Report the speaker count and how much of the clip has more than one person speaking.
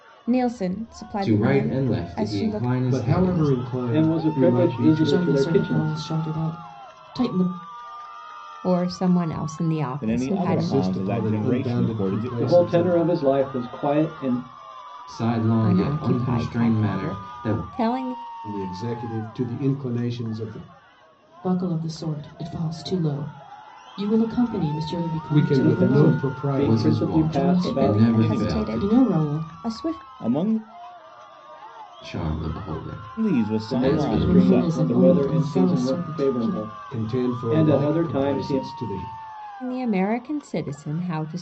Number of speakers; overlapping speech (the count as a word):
seven, about 49%